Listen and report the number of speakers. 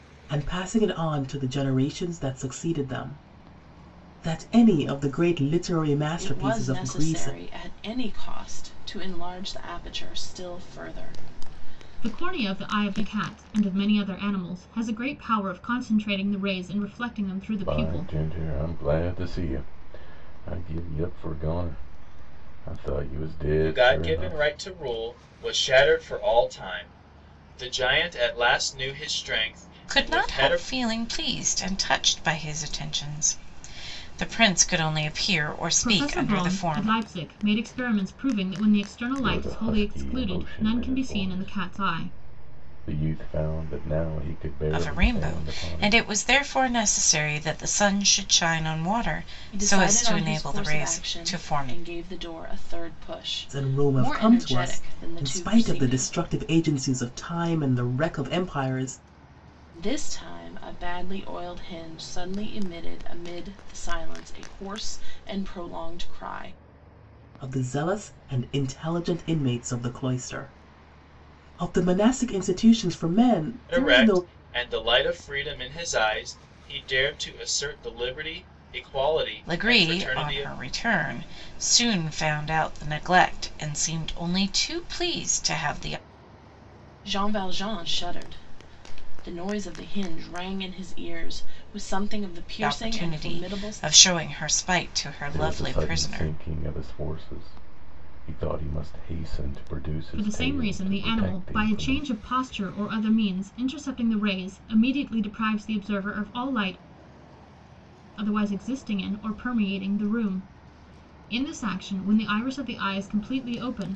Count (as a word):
six